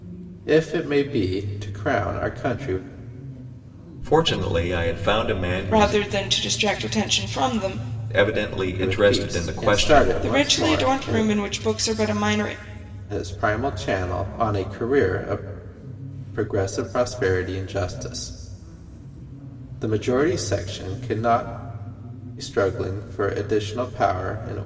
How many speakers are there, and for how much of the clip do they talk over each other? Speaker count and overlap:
three, about 11%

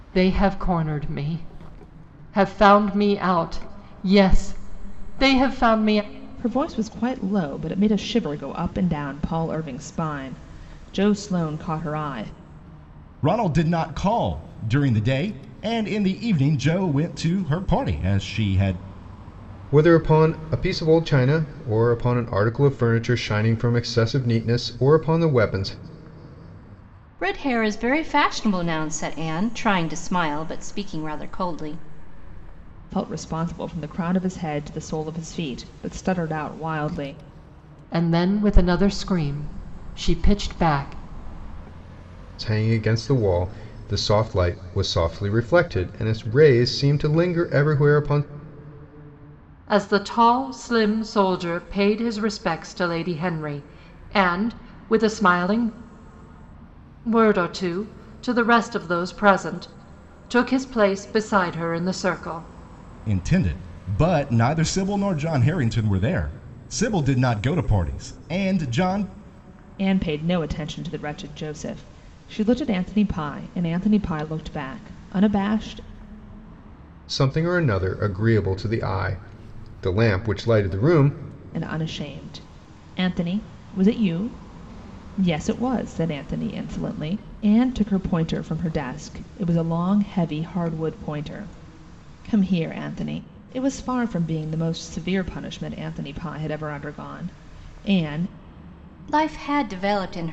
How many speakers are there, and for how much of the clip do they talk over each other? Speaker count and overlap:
five, no overlap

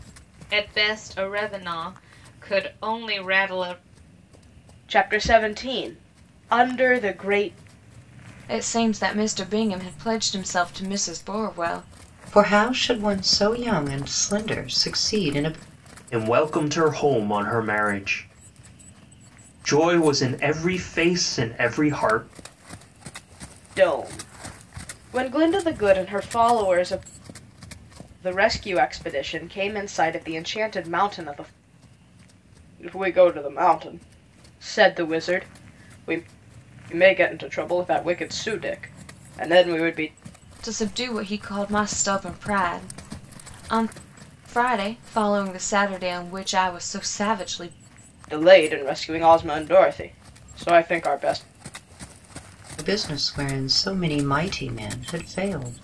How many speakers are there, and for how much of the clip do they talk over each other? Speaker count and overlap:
five, no overlap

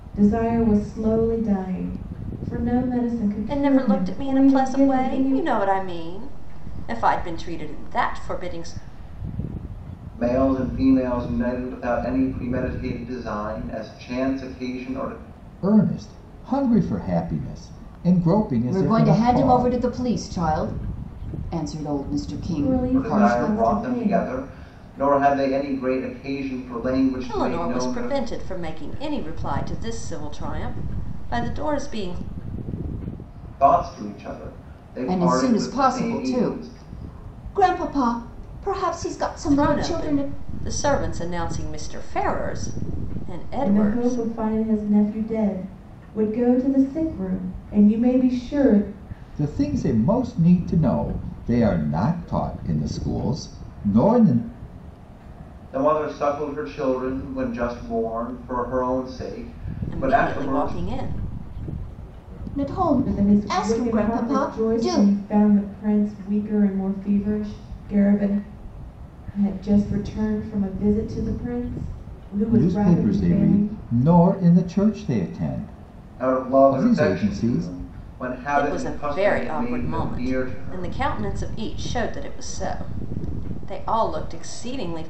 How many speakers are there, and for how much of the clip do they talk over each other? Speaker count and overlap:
five, about 20%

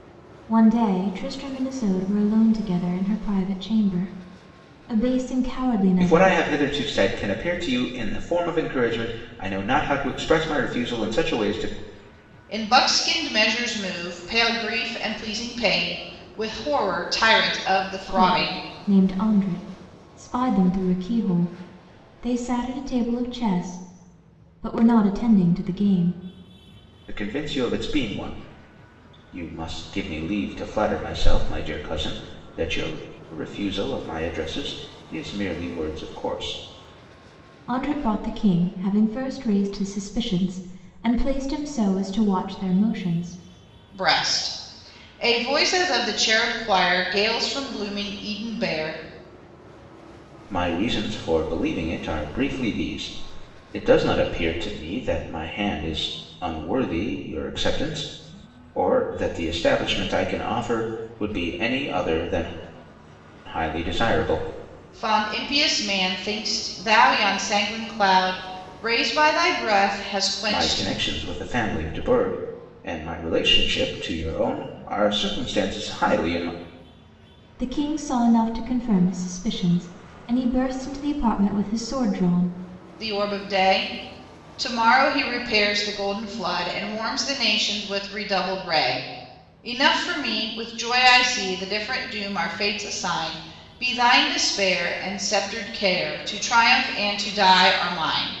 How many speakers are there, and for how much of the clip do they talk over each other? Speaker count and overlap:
three, about 2%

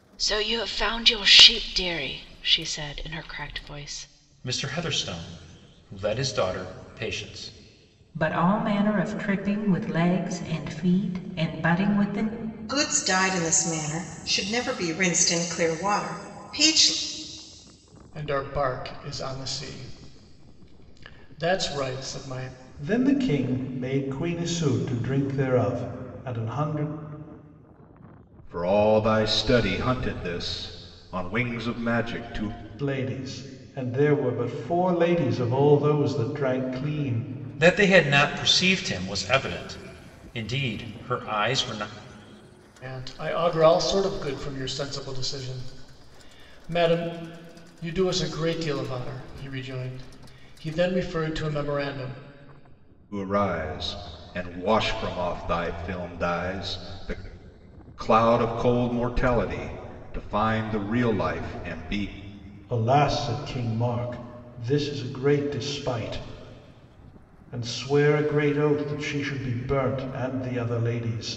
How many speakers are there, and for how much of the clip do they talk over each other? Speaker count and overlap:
seven, no overlap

